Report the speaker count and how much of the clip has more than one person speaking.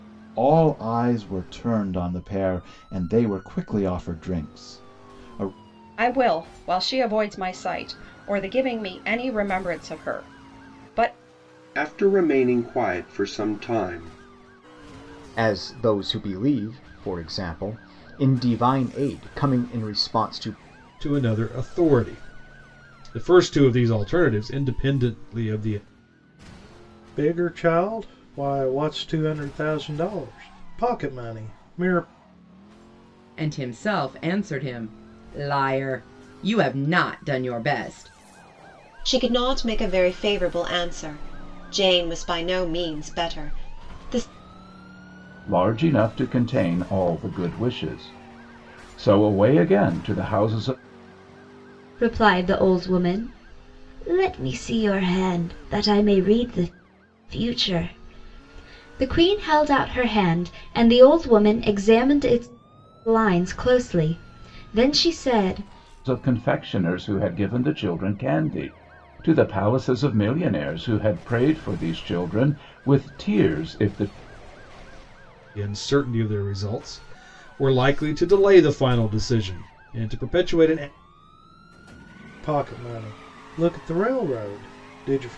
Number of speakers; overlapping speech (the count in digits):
10, no overlap